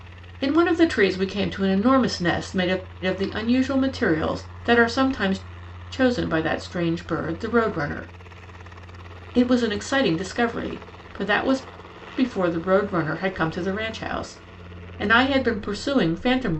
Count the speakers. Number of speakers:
one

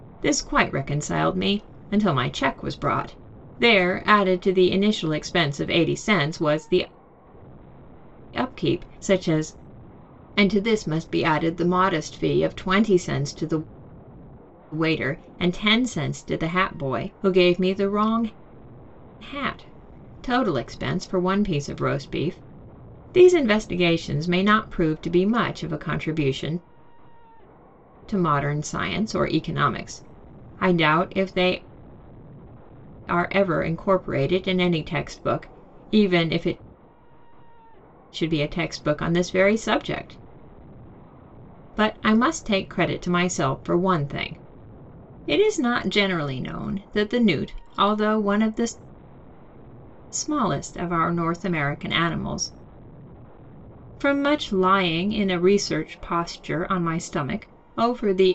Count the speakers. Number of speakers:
one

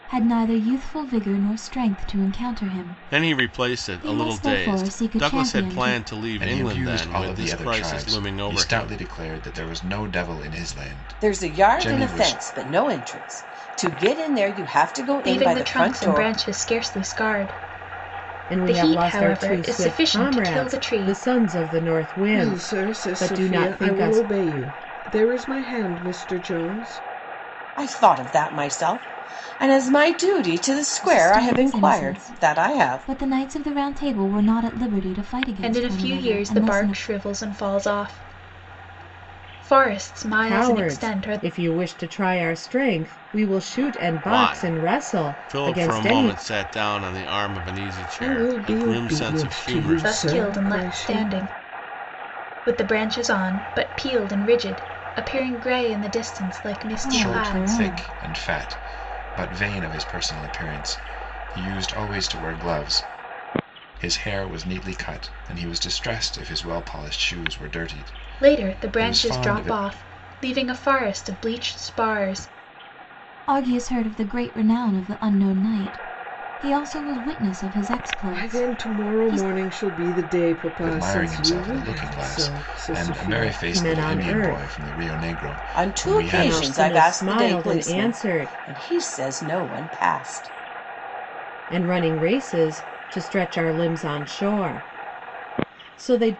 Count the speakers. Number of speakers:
seven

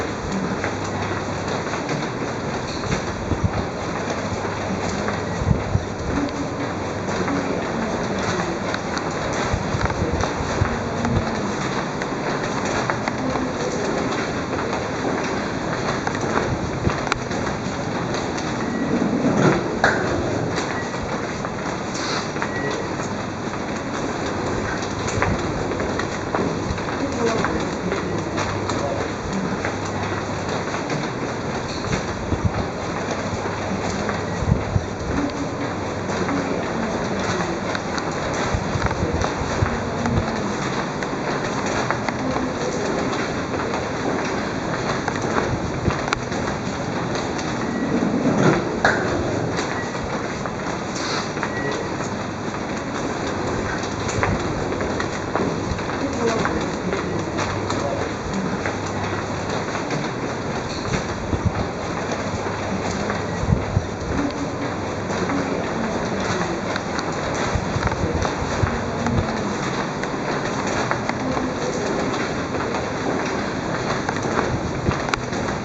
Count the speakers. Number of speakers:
zero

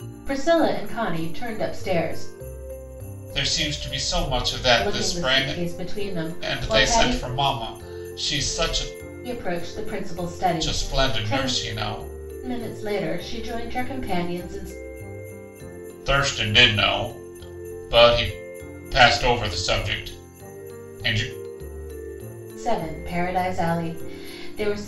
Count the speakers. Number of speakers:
two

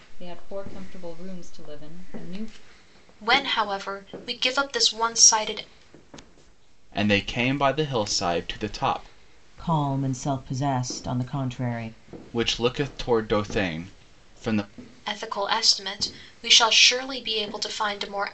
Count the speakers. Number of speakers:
four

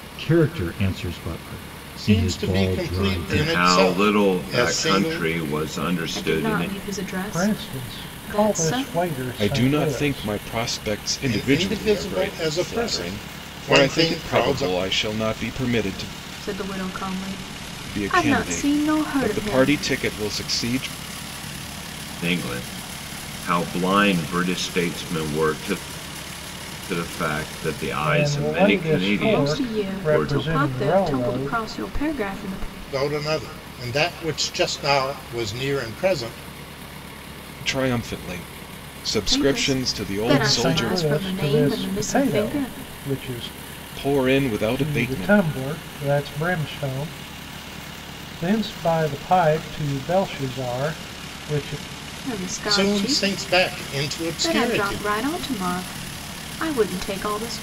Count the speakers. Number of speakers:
six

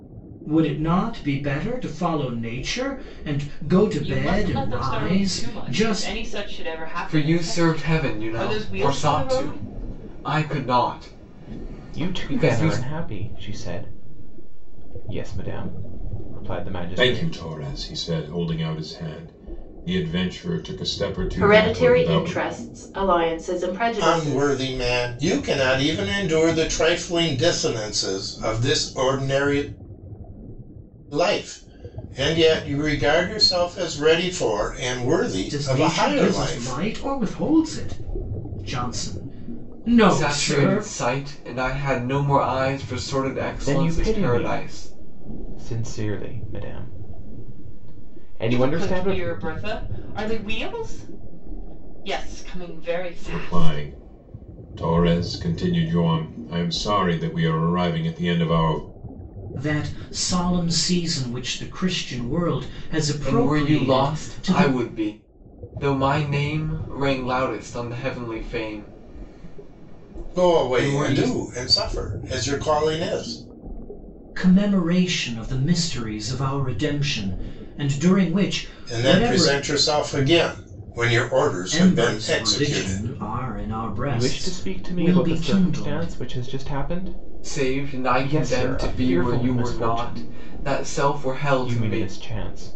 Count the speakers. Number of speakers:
seven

